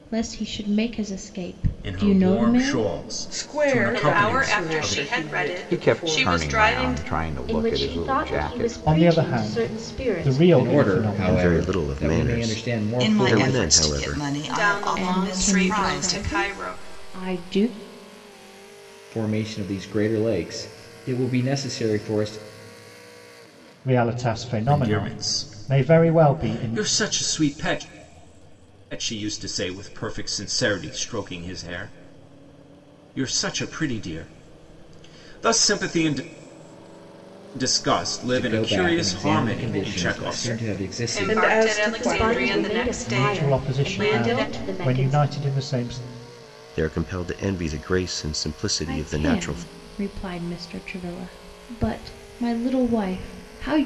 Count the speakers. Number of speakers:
ten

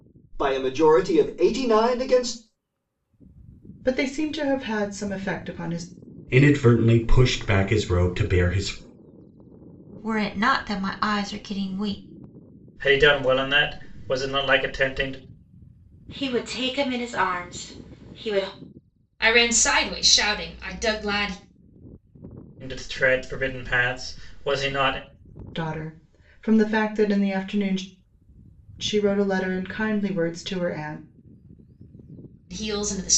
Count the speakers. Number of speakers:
seven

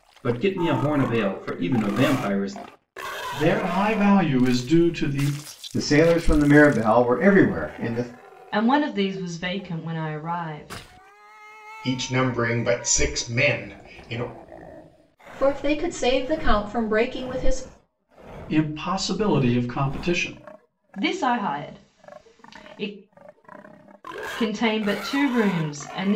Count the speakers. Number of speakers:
six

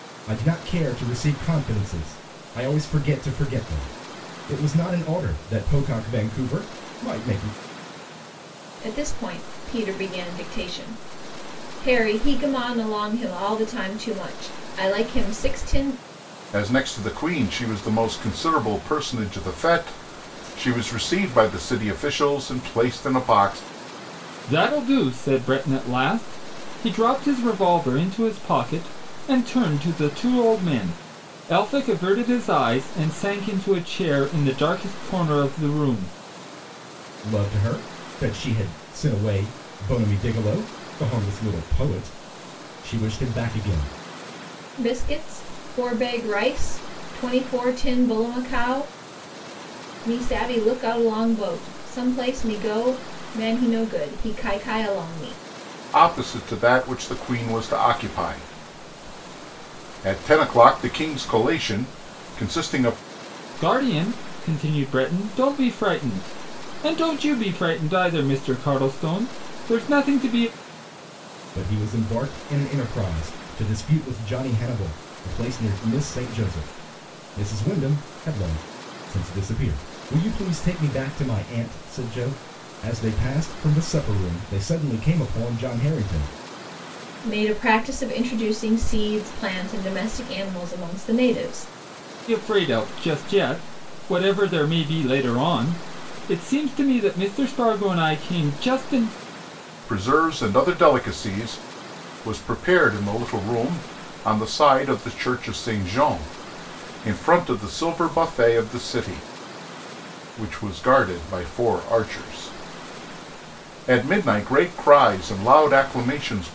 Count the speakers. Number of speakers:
four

